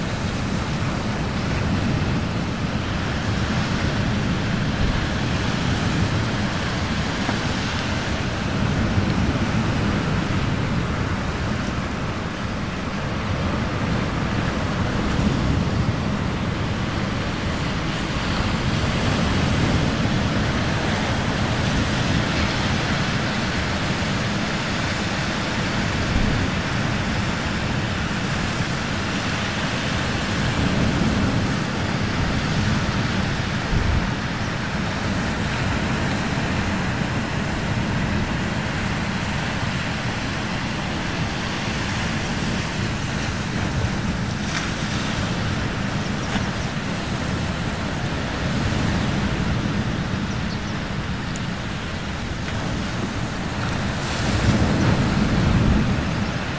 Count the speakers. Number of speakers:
zero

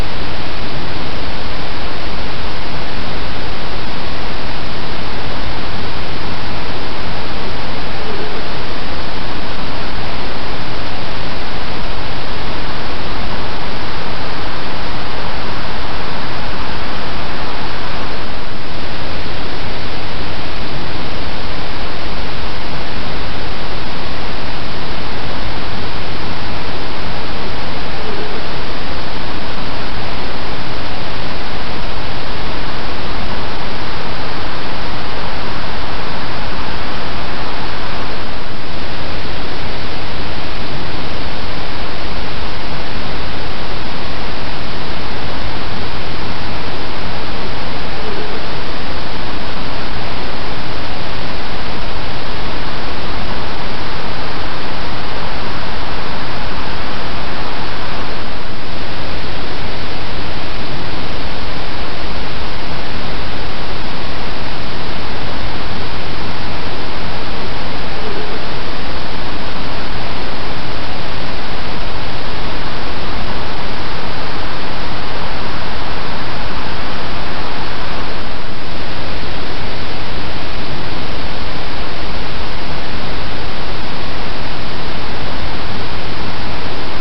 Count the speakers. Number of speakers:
zero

